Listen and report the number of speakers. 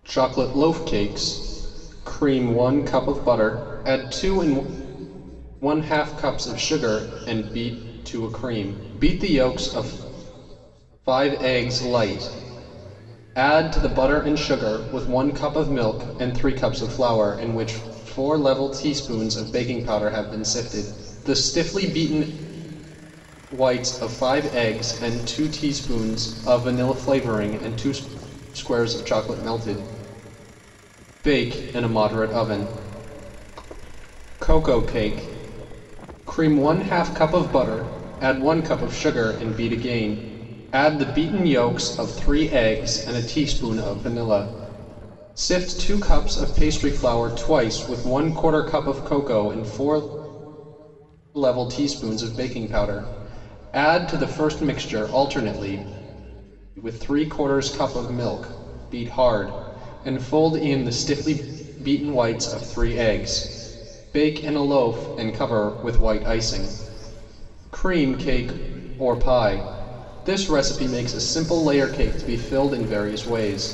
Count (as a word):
one